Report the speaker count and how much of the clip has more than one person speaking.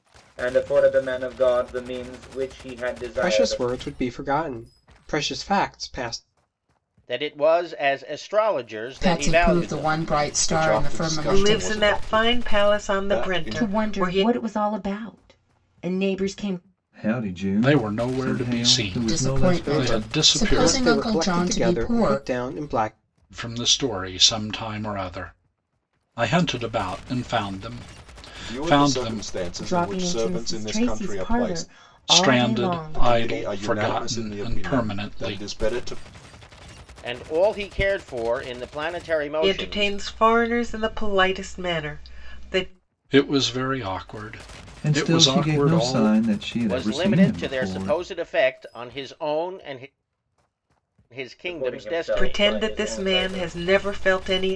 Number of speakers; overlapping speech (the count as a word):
nine, about 40%